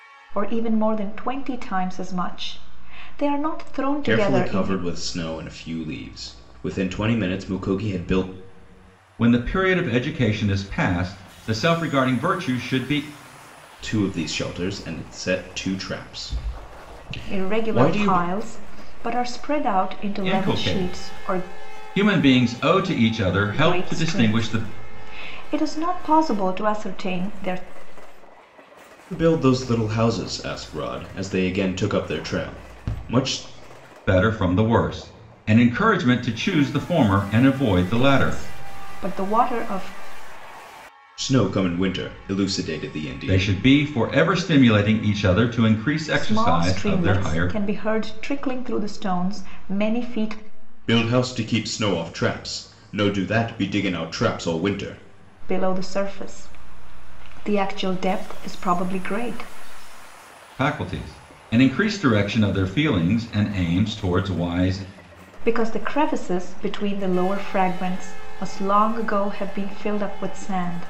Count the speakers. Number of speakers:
three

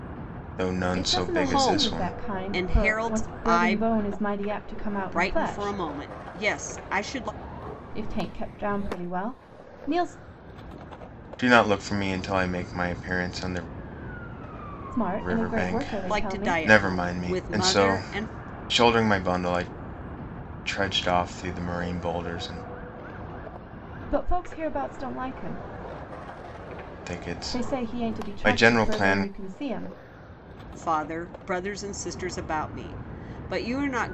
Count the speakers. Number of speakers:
three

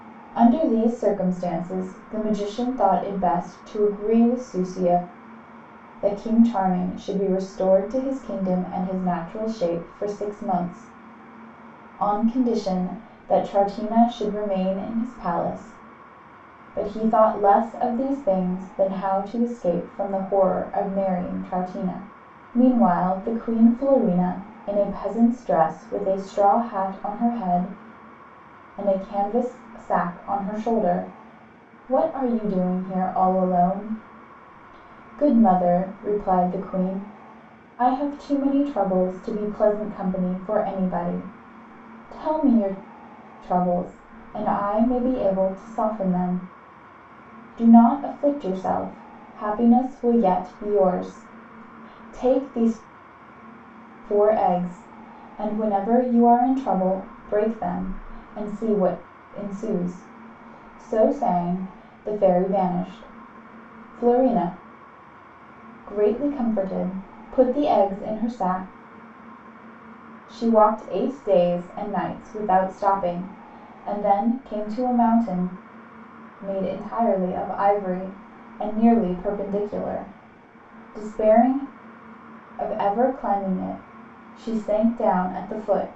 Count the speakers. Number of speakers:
one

